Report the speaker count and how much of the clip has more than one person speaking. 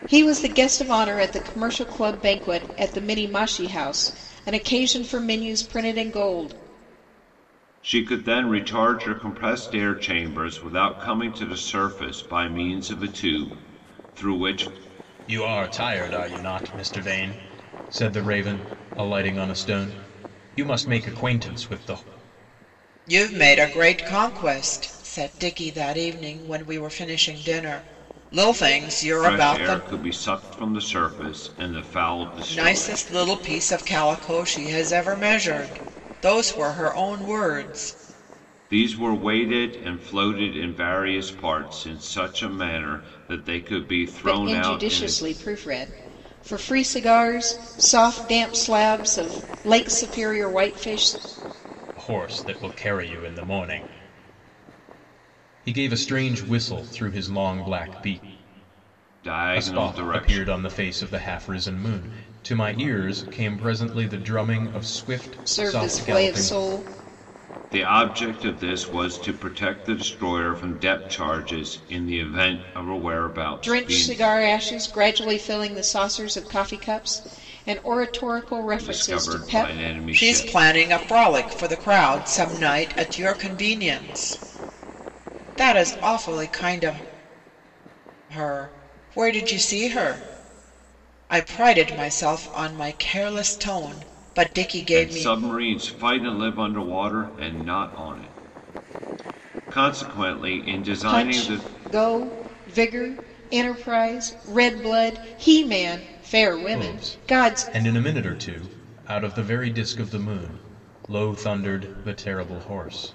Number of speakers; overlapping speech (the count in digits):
4, about 8%